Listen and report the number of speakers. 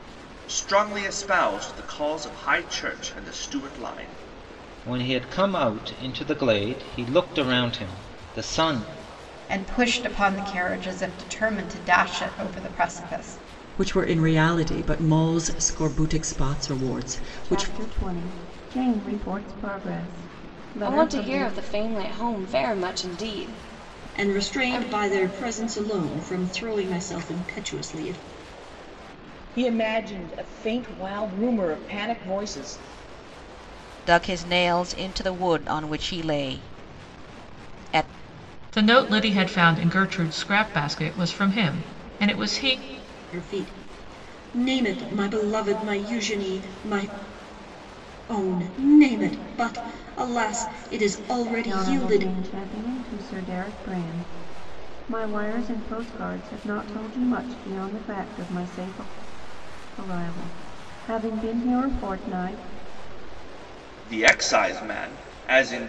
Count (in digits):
10